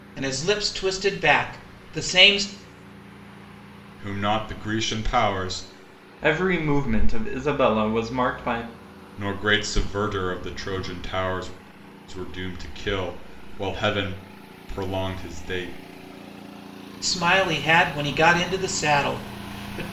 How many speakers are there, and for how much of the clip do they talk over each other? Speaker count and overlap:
3, no overlap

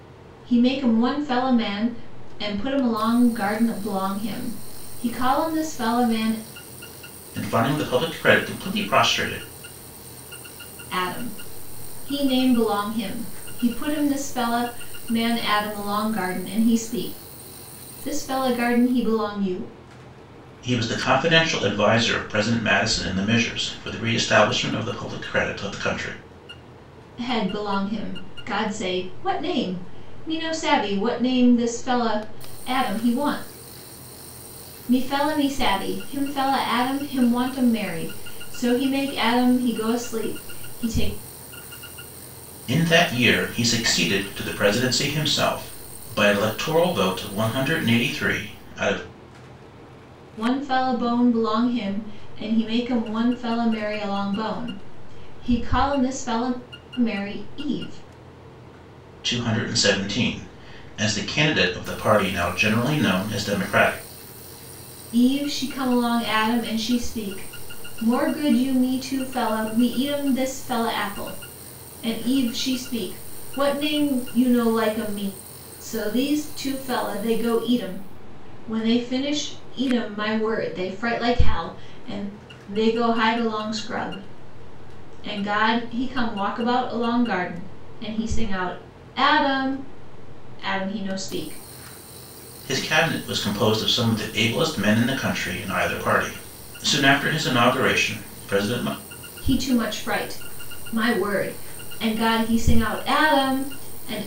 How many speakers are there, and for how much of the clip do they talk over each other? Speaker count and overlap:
2, no overlap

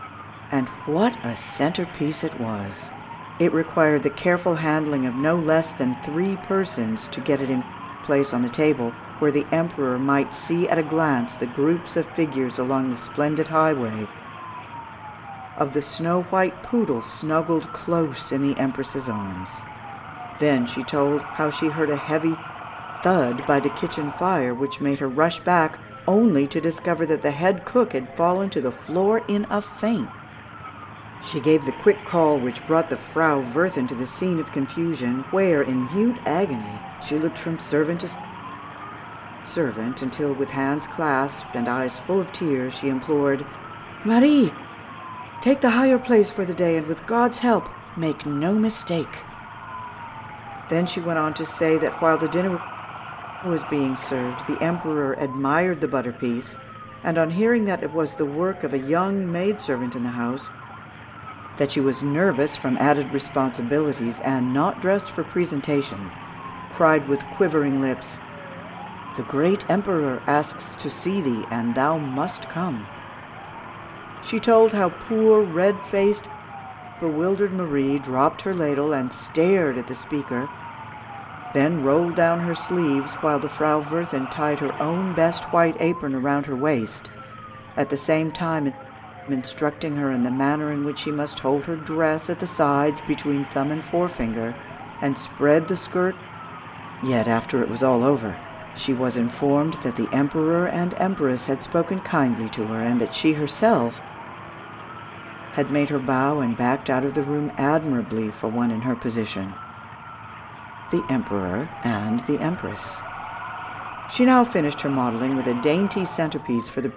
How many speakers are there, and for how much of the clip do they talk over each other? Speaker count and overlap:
1, no overlap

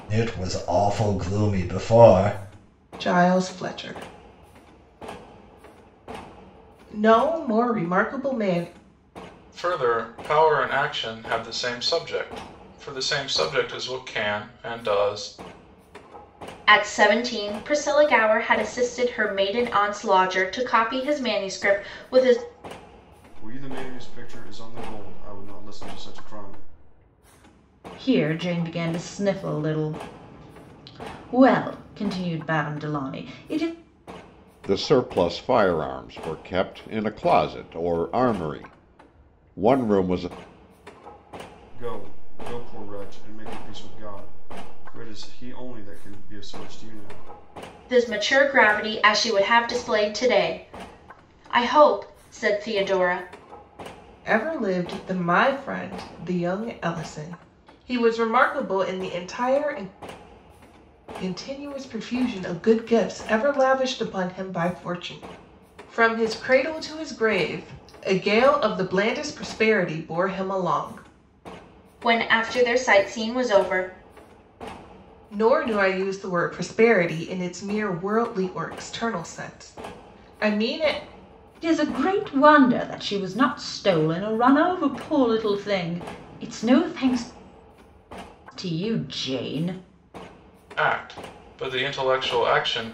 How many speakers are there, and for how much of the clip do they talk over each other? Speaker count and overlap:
7, no overlap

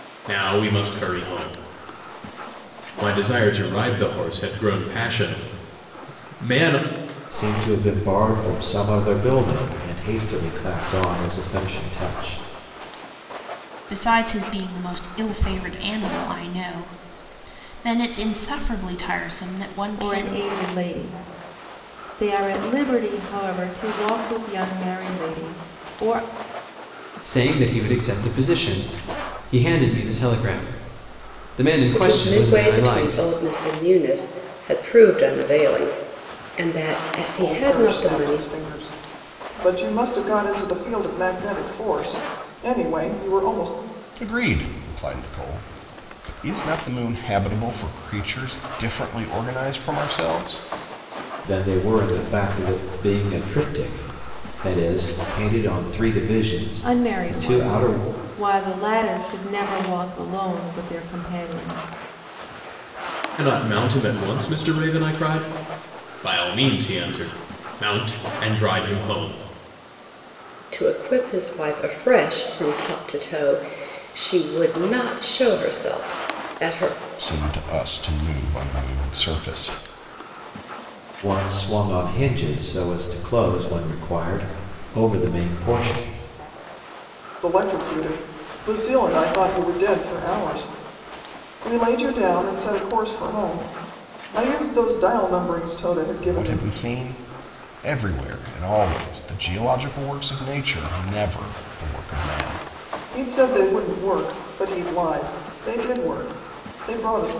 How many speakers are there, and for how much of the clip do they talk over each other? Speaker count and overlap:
8, about 4%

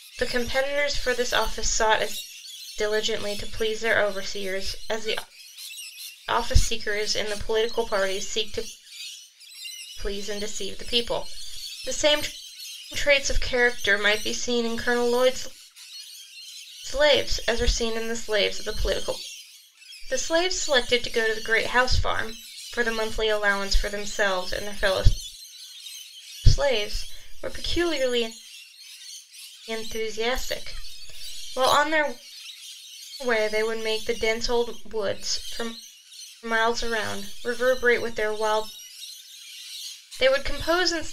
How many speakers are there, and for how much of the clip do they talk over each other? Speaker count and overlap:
1, no overlap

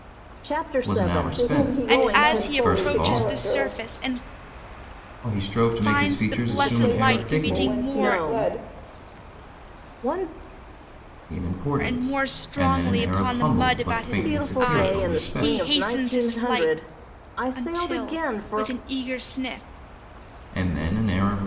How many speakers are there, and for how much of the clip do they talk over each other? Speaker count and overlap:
4, about 56%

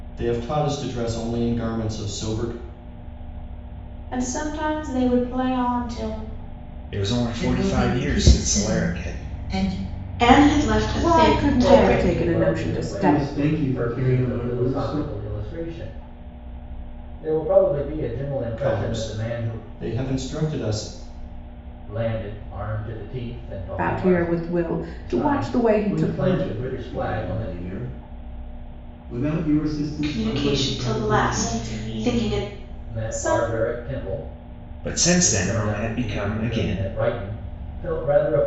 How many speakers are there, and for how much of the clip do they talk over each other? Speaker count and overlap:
8, about 39%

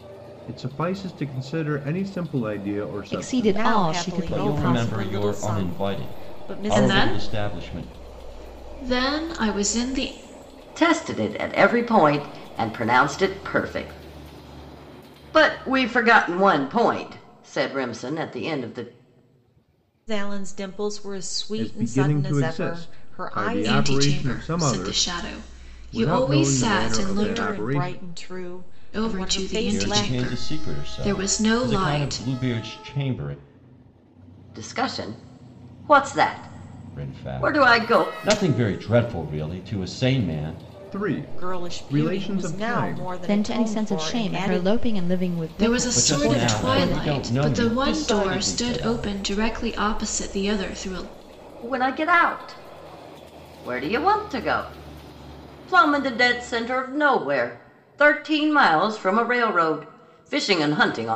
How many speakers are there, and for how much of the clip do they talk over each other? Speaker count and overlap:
6, about 36%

